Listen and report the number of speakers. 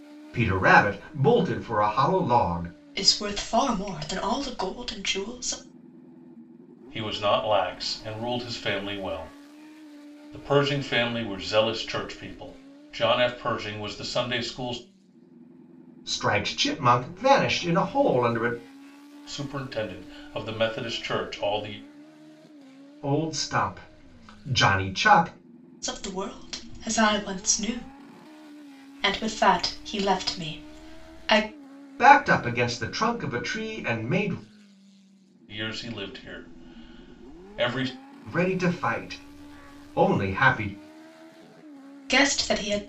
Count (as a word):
three